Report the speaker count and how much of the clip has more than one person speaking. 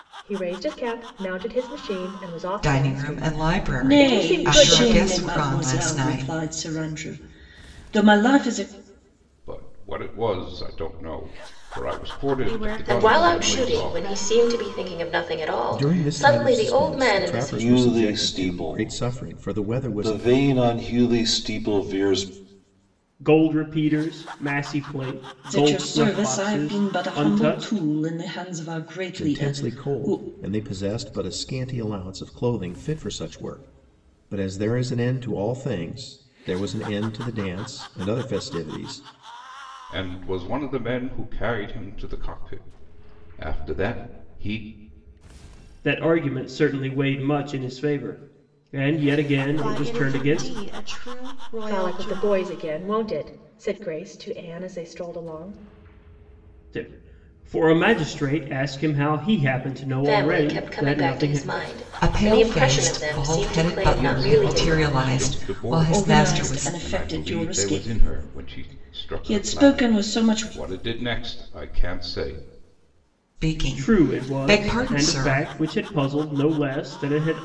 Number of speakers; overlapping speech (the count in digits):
9, about 35%